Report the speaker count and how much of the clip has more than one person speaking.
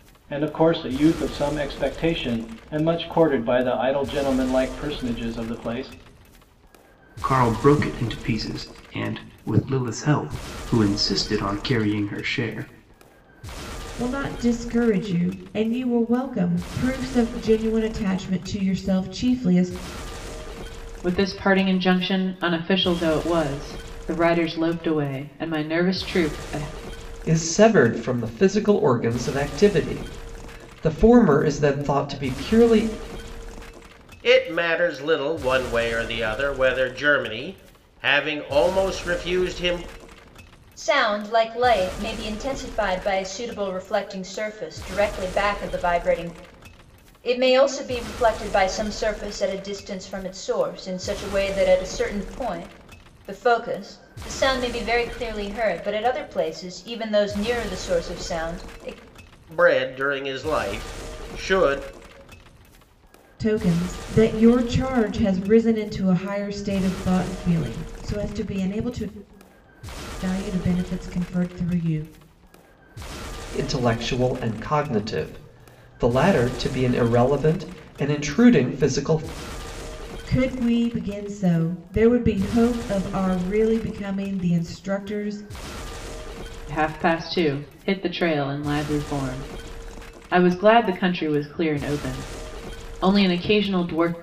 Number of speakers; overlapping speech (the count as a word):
seven, no overlap